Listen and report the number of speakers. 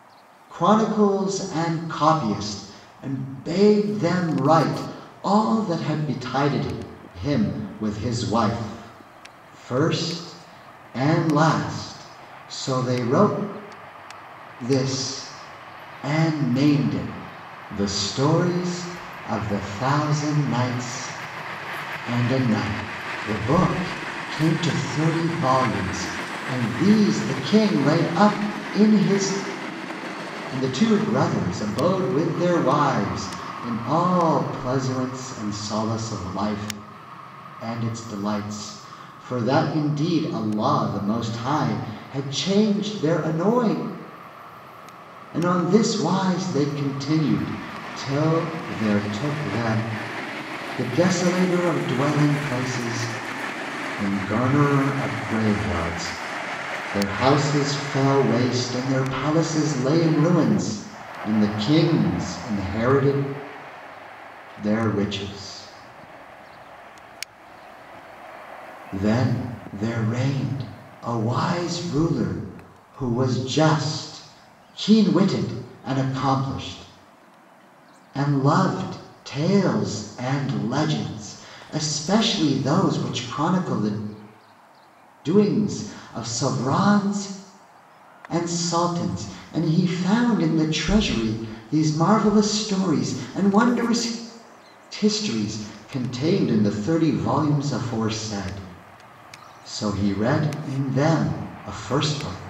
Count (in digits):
1